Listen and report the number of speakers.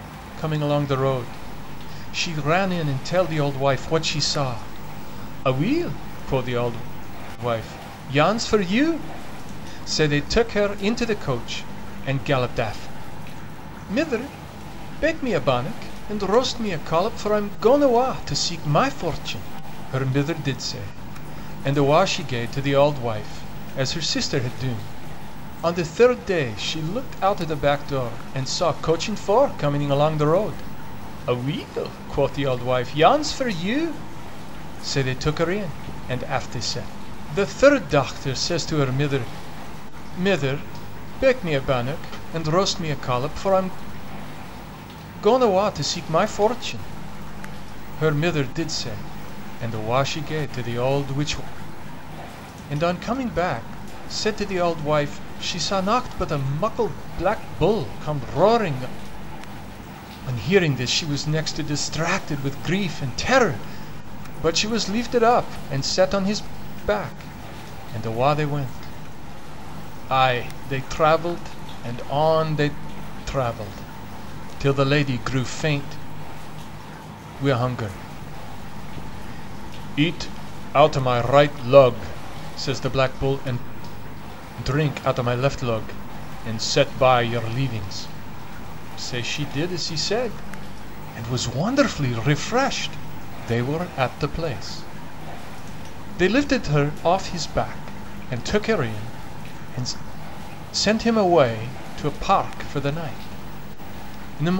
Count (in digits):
1